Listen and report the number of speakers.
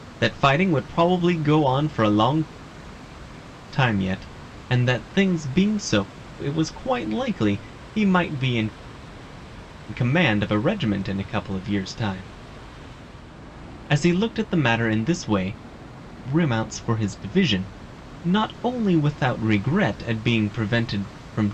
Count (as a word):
one